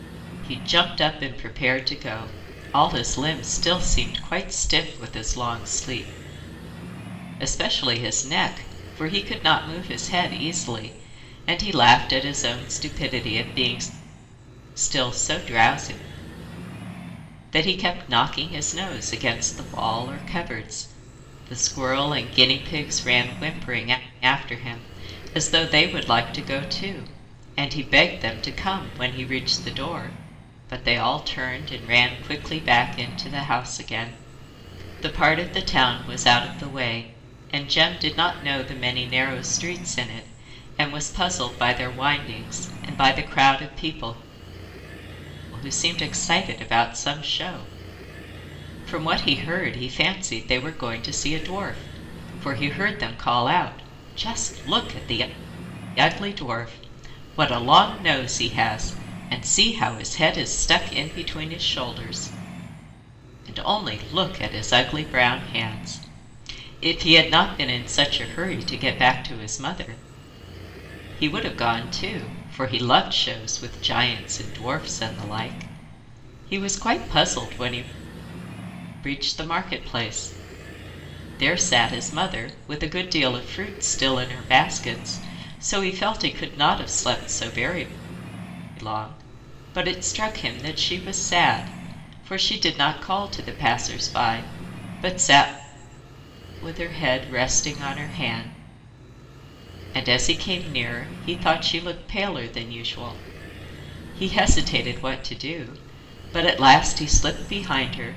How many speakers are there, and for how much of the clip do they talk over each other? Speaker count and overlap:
1, no overlap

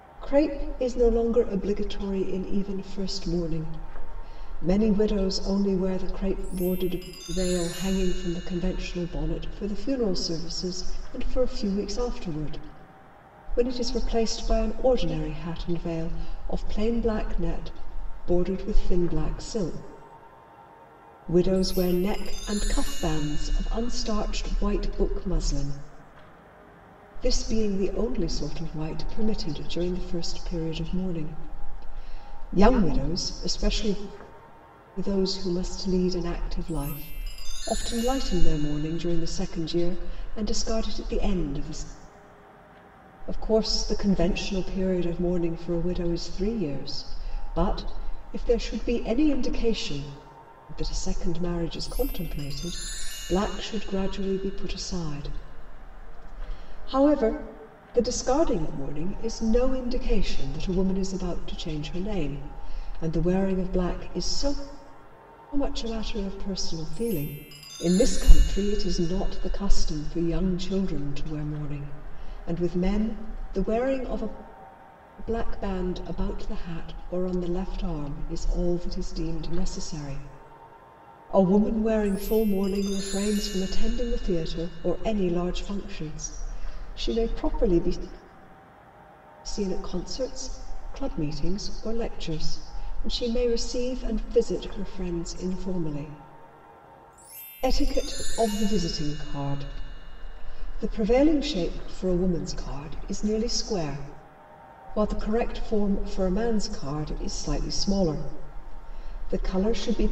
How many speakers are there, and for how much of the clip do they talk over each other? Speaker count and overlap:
1, no overlap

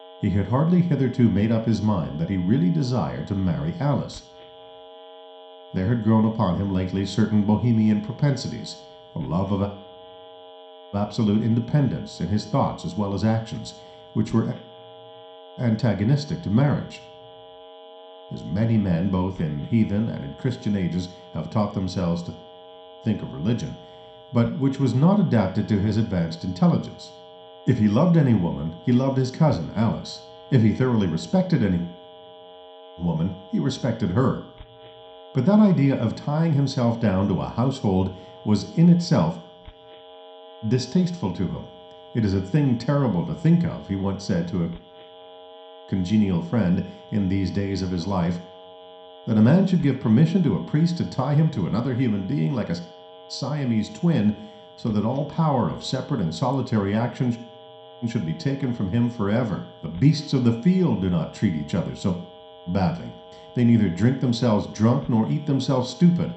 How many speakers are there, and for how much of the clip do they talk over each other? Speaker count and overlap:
1, no overlap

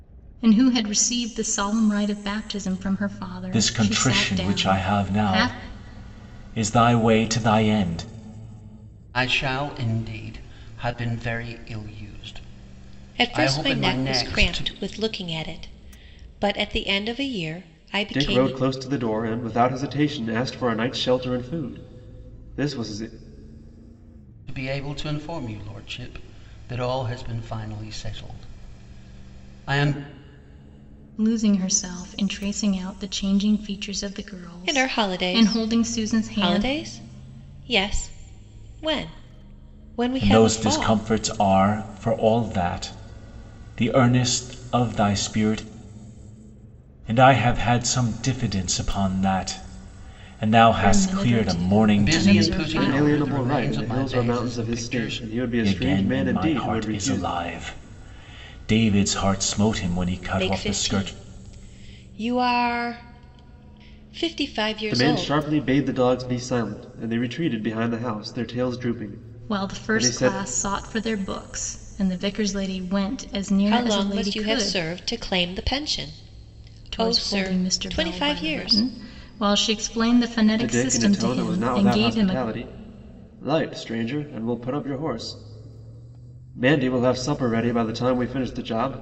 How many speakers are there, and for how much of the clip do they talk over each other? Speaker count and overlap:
5, about 24%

